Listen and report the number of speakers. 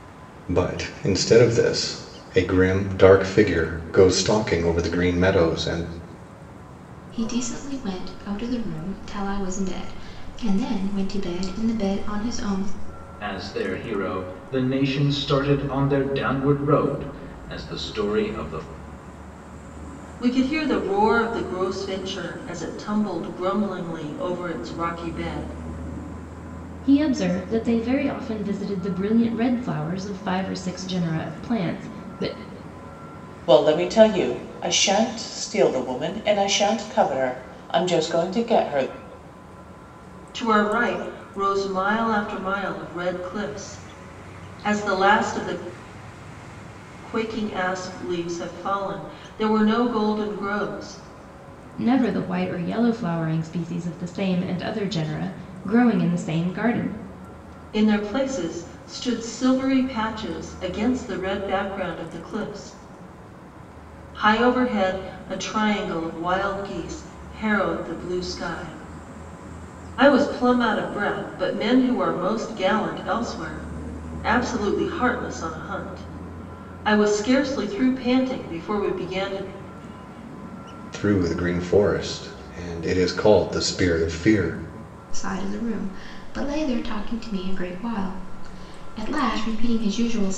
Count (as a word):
six